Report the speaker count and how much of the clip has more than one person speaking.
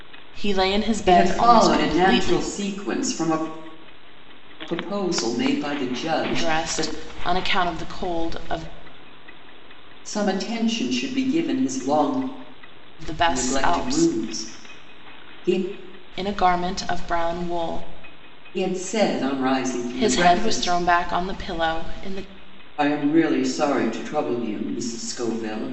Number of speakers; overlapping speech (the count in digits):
2, about 15%